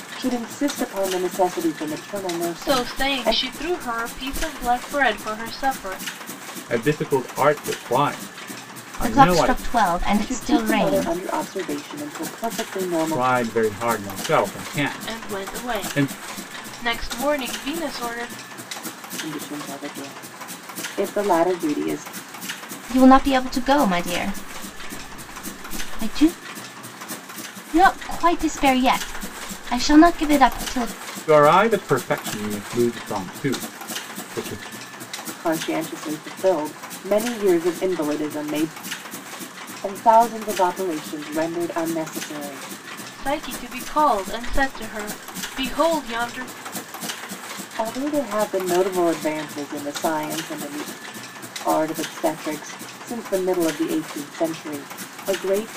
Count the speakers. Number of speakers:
4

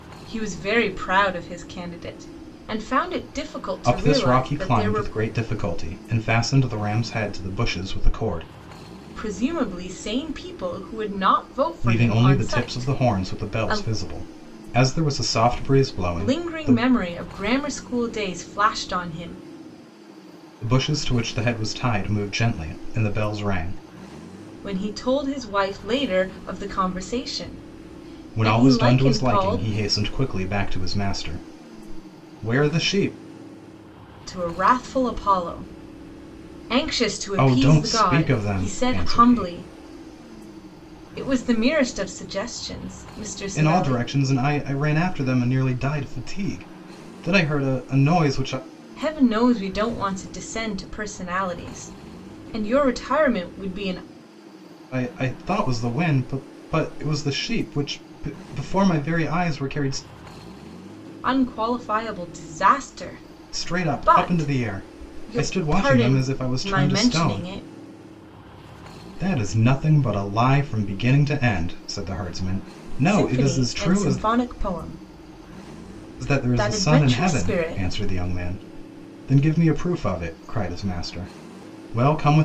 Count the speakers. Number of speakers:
2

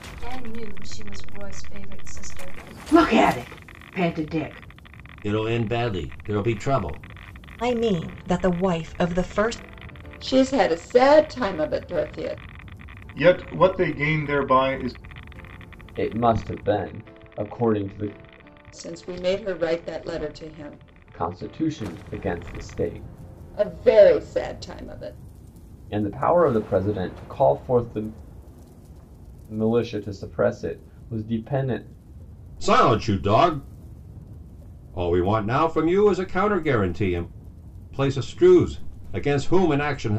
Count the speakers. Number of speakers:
7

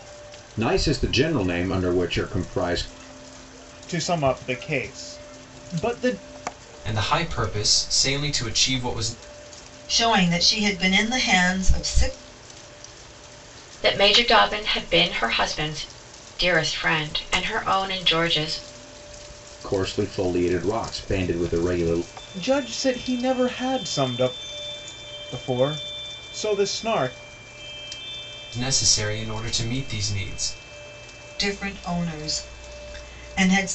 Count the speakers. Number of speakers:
5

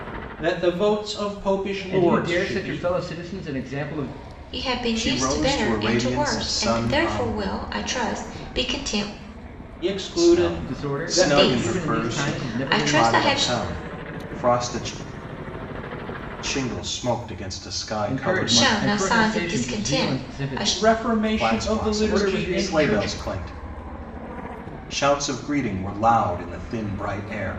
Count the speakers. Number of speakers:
4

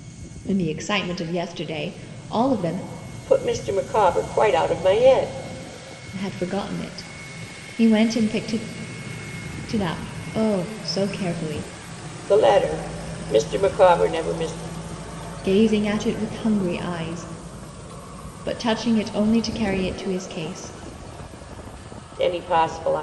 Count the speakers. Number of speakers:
2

